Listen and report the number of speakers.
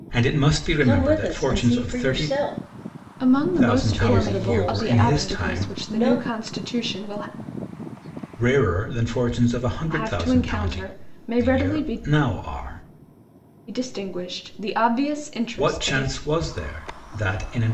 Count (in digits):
3